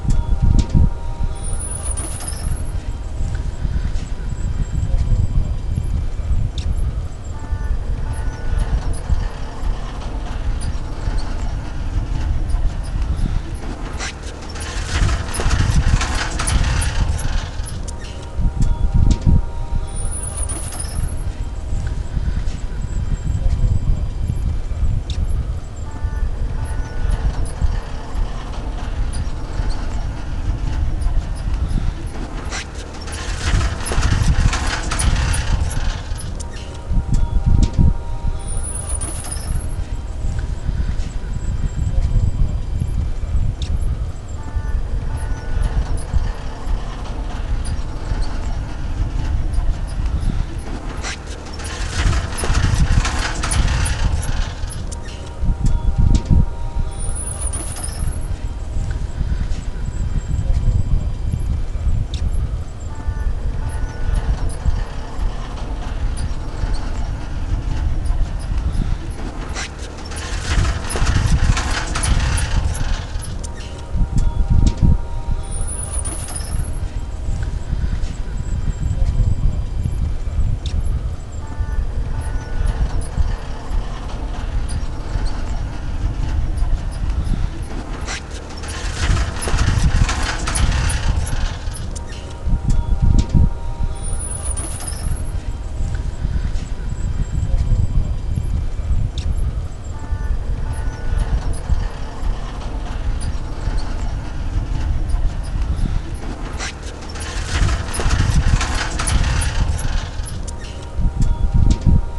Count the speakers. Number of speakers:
0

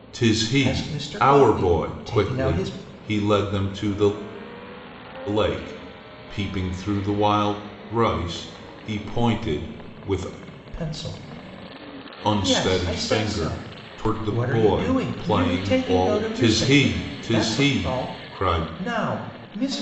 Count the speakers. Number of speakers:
2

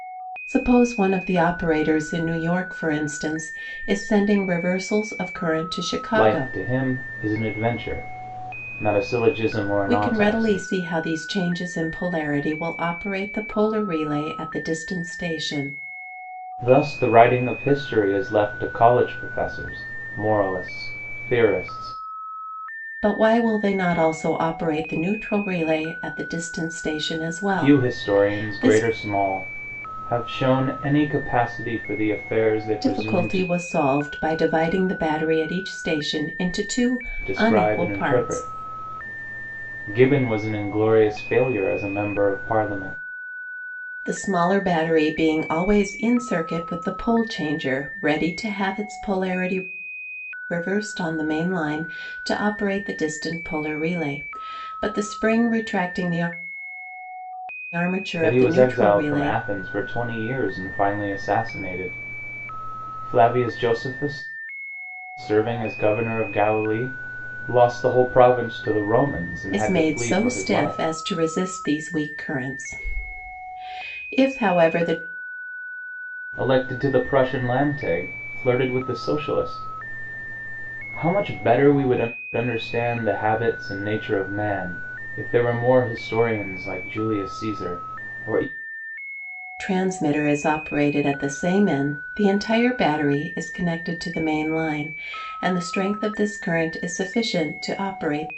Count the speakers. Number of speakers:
2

